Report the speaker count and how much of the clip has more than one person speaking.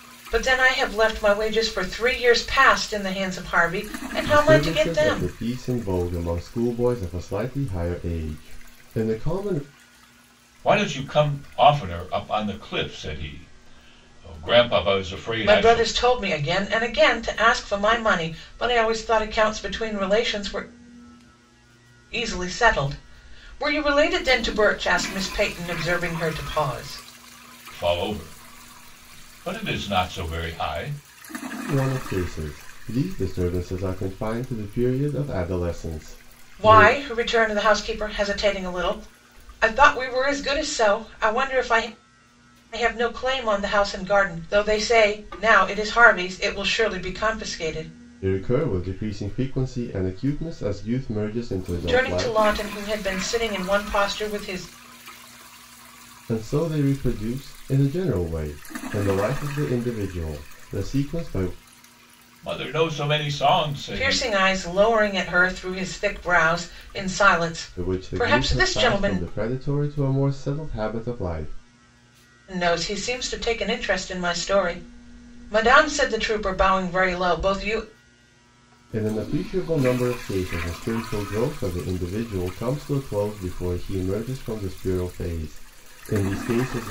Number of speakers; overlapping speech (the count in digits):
3, about 5%